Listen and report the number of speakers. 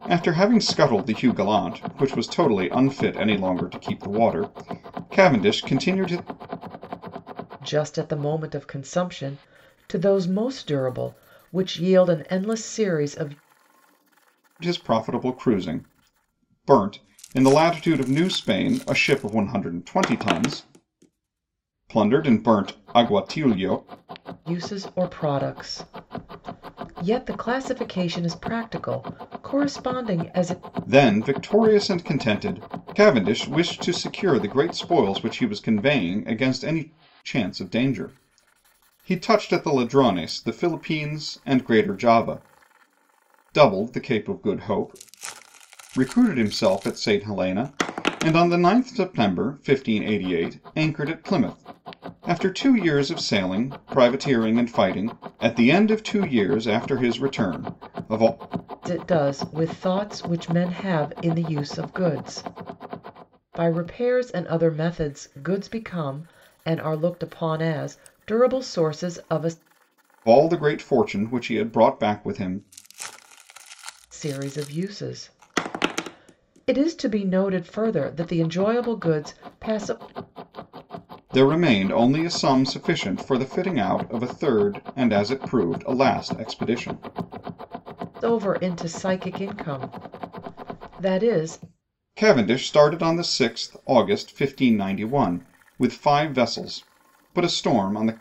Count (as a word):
two